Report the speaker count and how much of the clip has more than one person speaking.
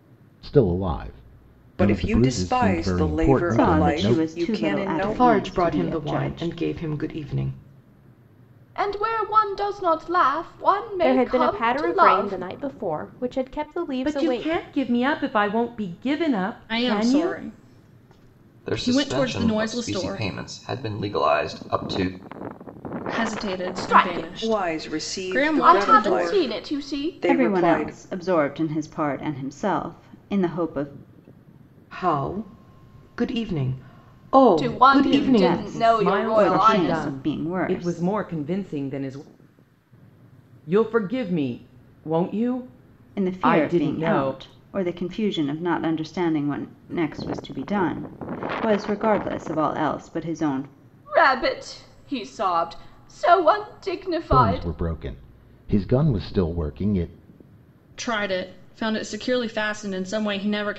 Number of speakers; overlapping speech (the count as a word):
nine, about 31%